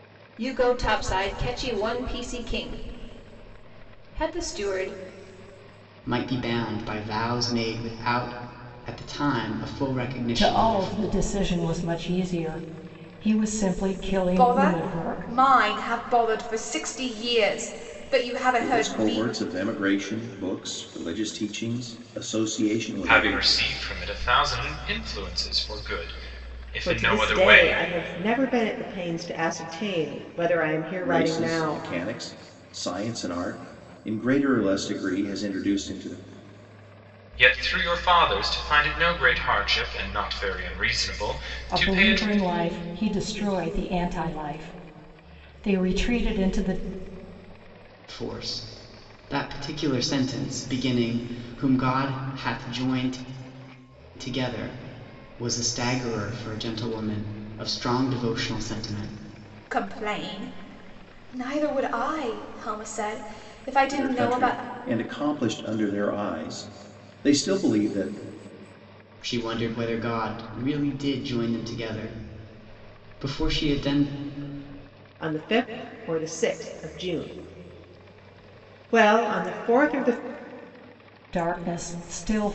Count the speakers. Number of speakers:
7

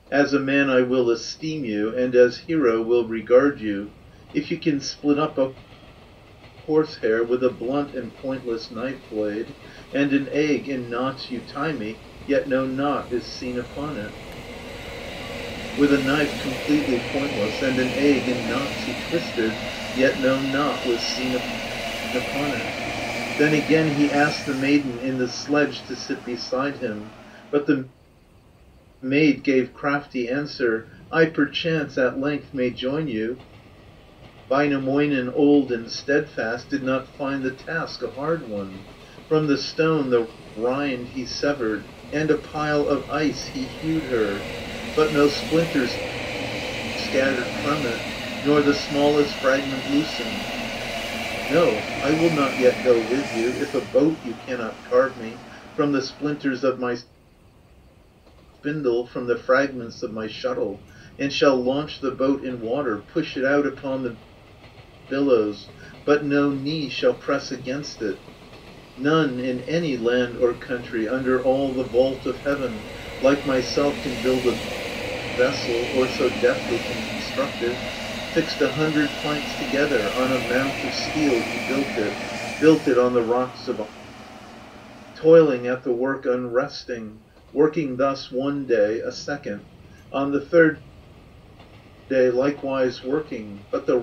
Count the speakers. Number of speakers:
1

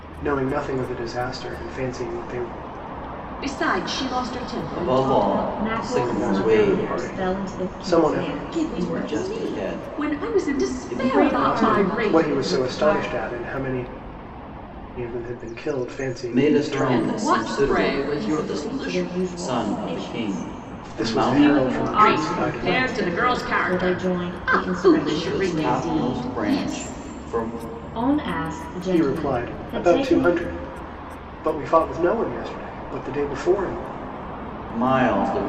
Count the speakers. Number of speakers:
4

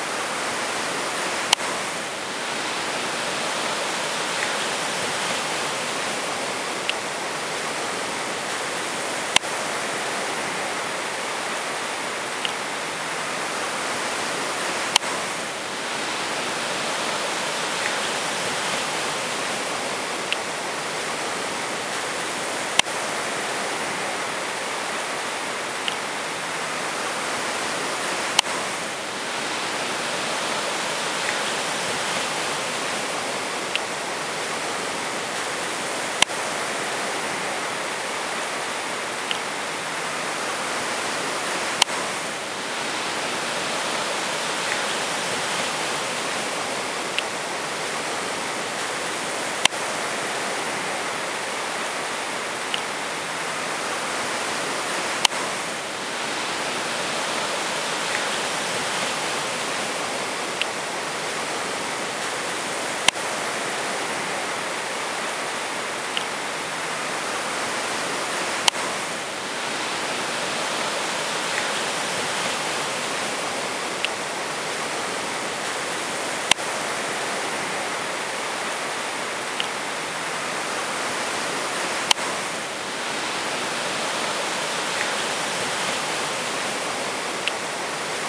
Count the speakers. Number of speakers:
0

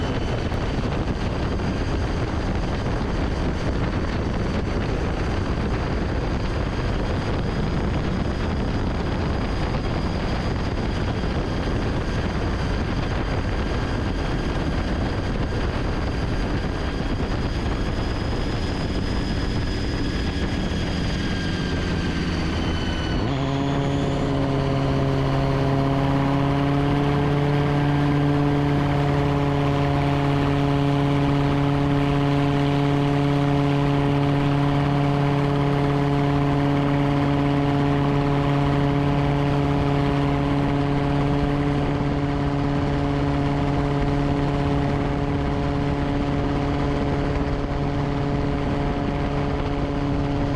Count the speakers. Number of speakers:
0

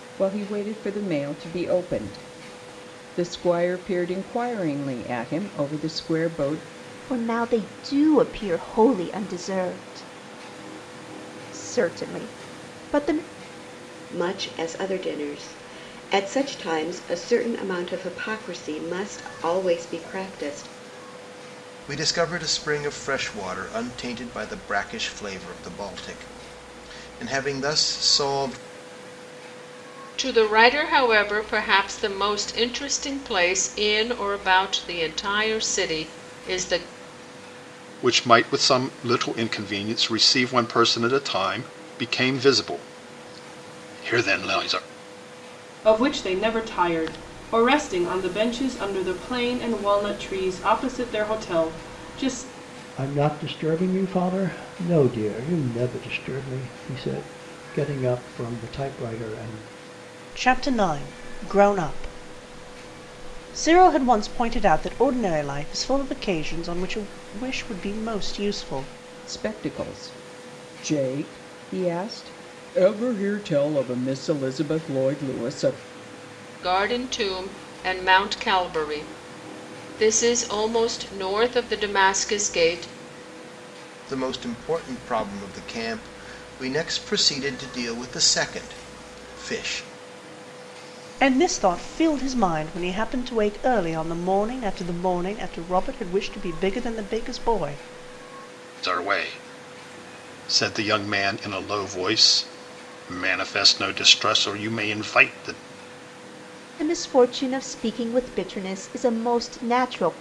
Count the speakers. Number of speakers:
9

